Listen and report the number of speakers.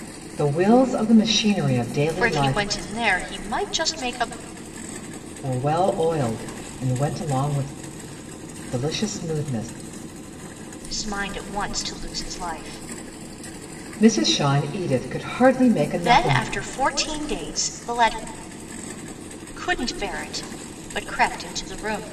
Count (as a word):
two